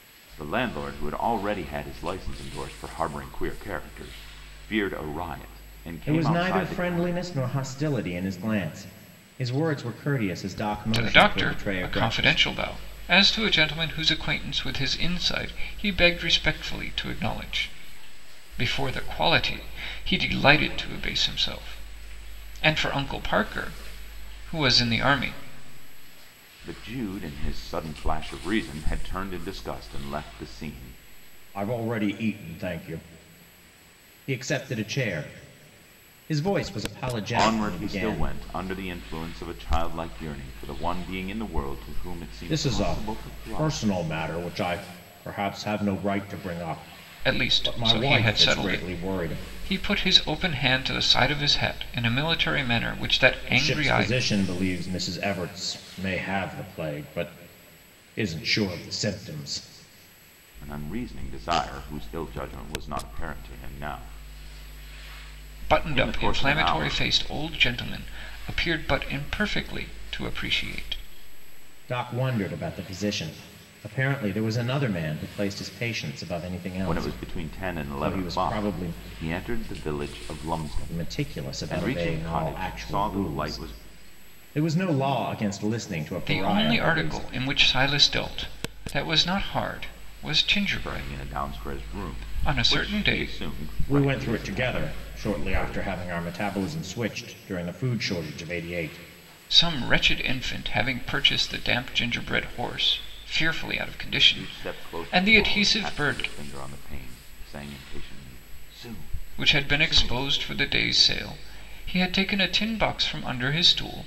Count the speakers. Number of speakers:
three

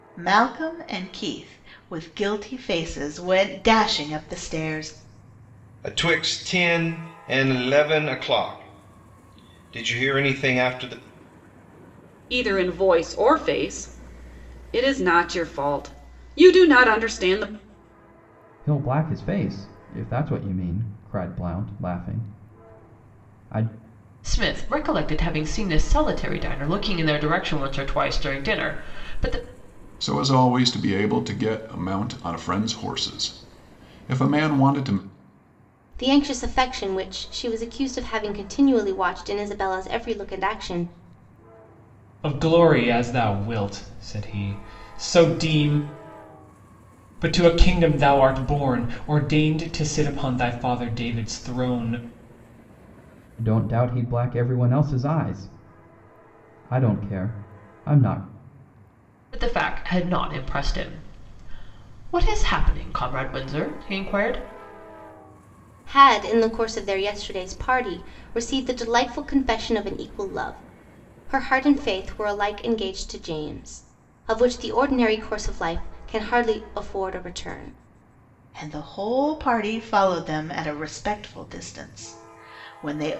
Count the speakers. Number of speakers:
eight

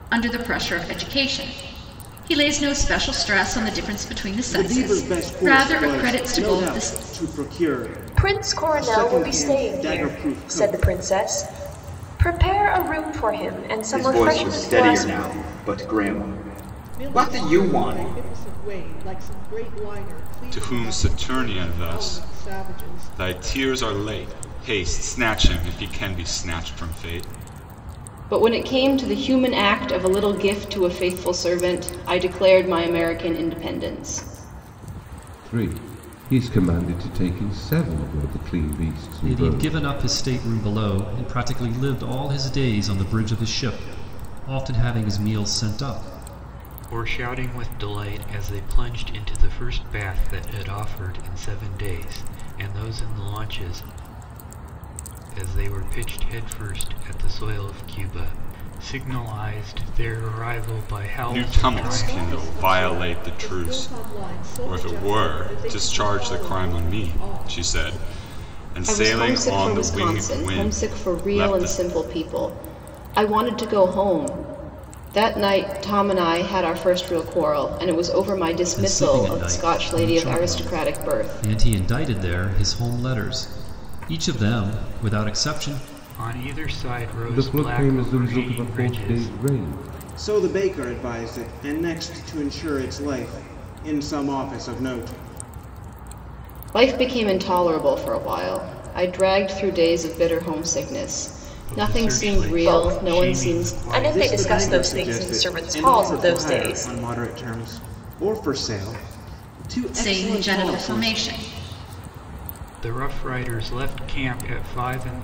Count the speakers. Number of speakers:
ten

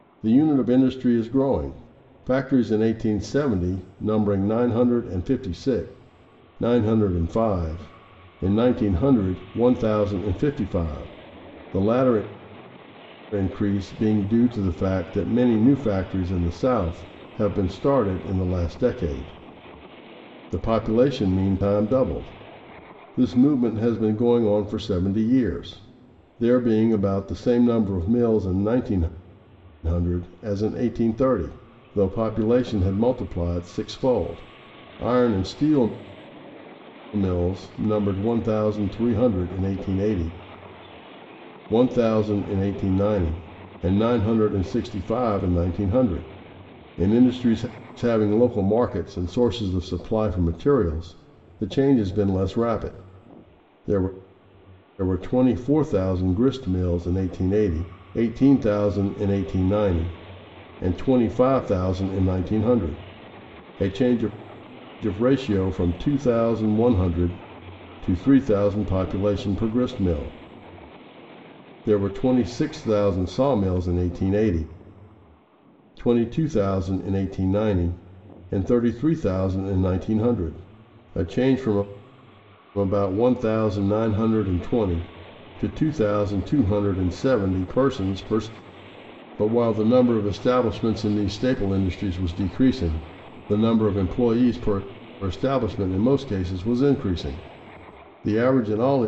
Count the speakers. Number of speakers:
one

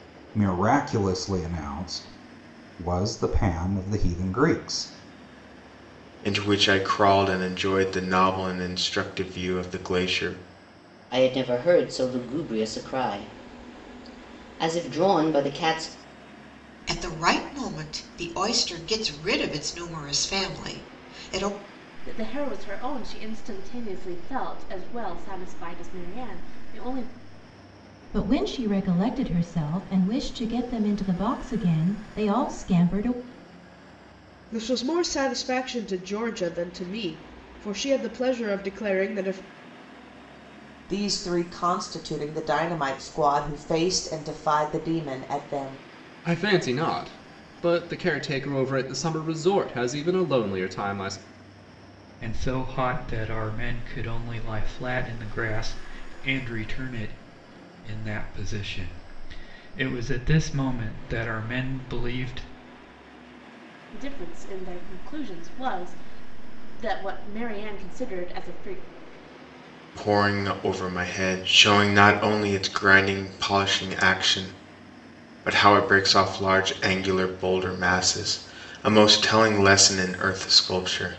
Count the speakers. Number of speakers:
ten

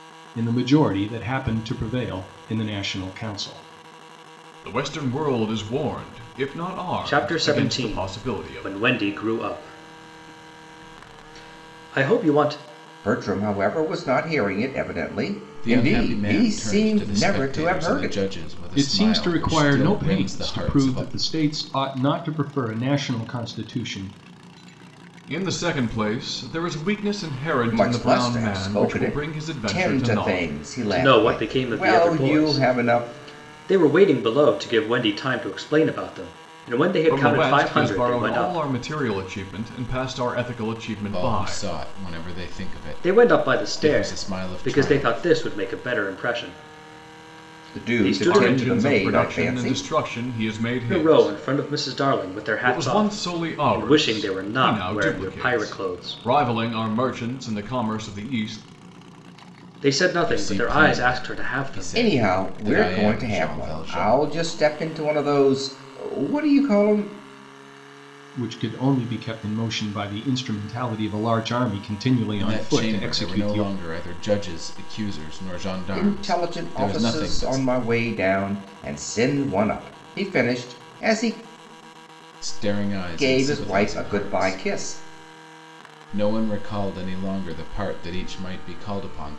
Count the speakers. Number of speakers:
five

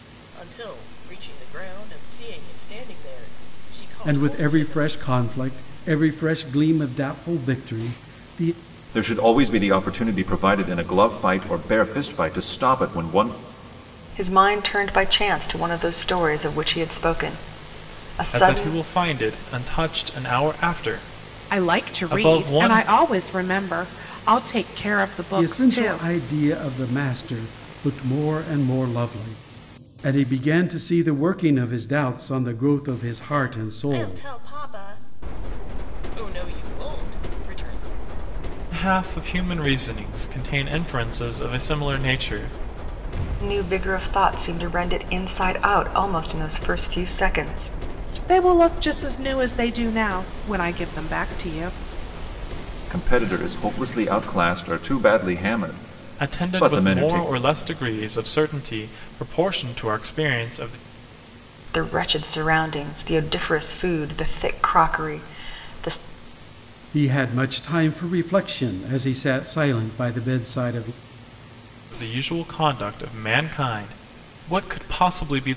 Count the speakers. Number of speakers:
six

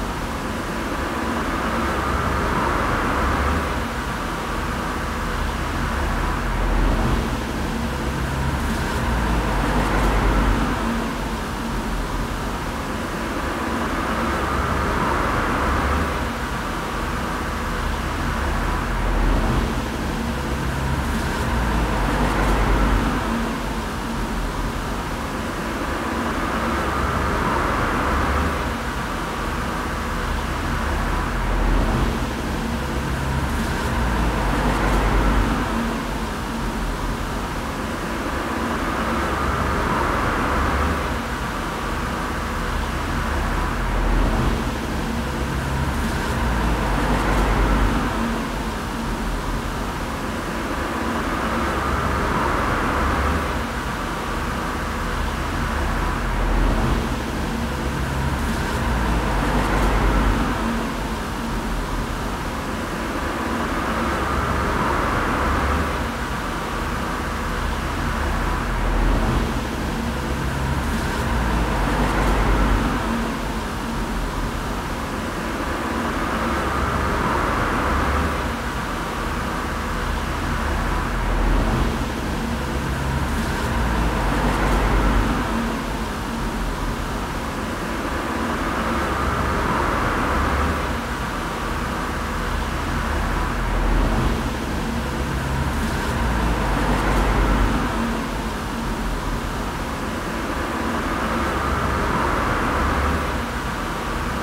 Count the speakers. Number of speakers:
zero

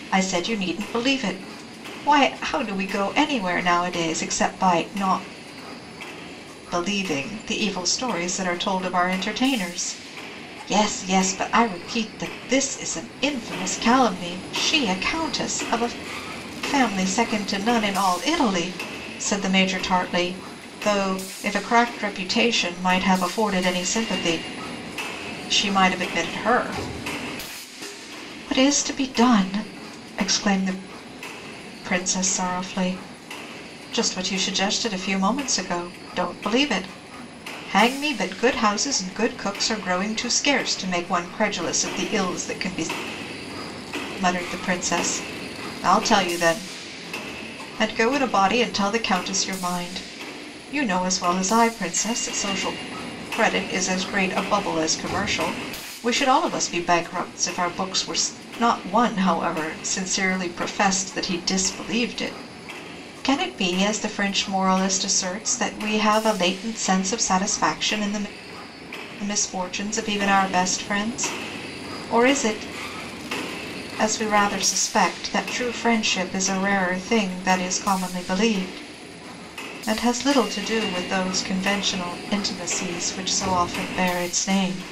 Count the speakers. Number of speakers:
one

